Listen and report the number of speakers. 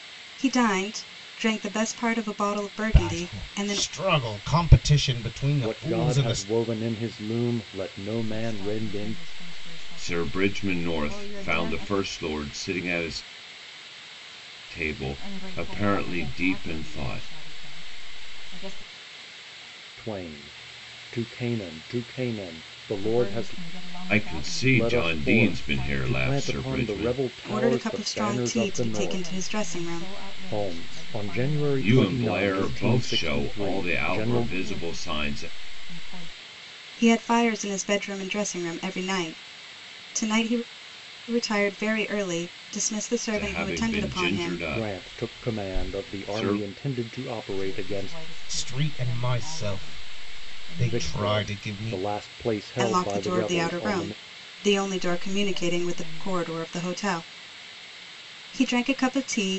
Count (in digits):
5